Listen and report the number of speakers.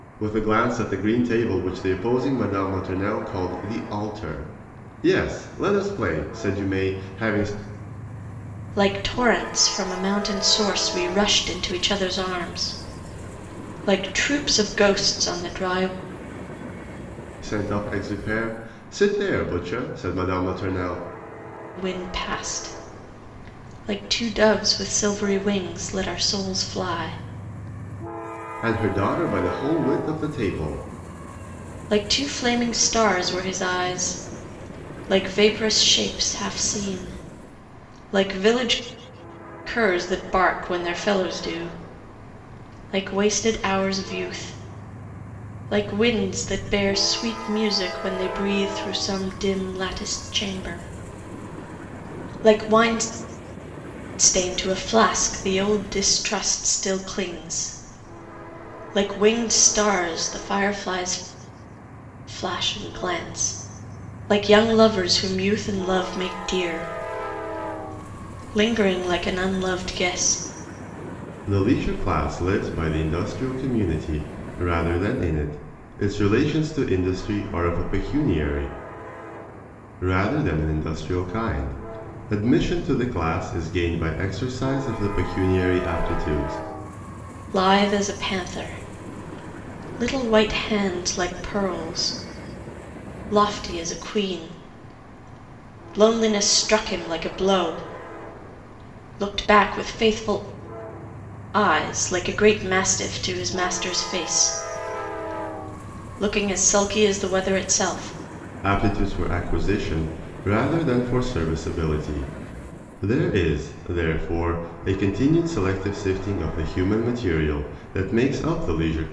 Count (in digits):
2